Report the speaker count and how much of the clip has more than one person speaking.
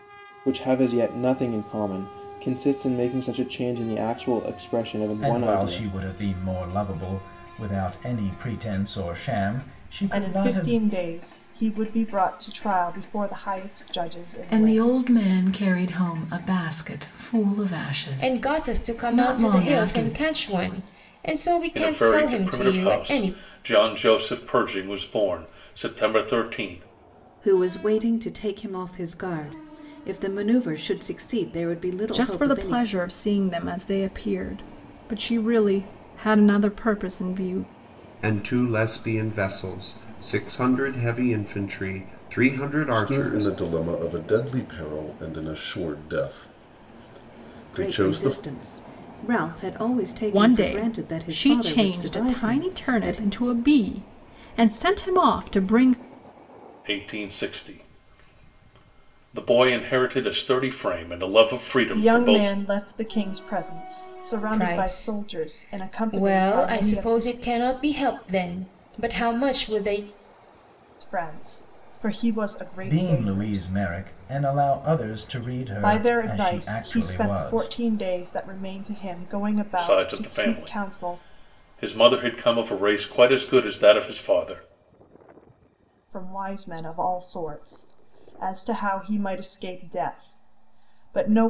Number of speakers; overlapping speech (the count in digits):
10, about 20%